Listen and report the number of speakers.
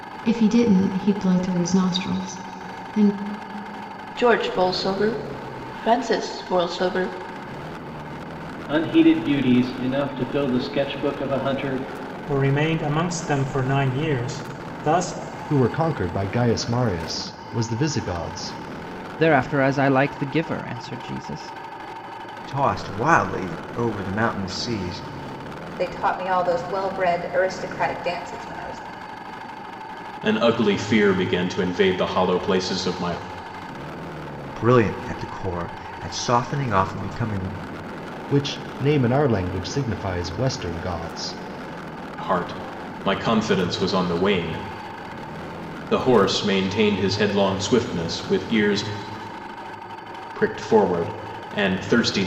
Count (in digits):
9